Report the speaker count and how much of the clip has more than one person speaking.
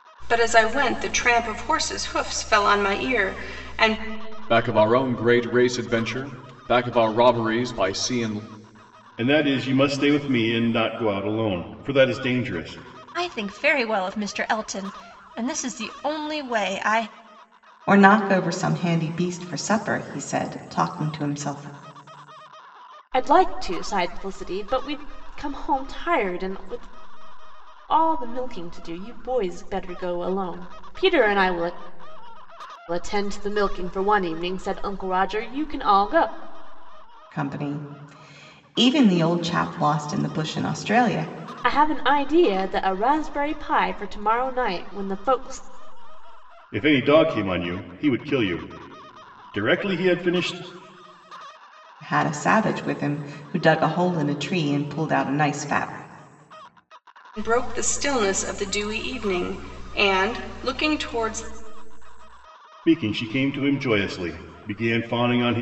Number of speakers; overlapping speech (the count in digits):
6, no overlap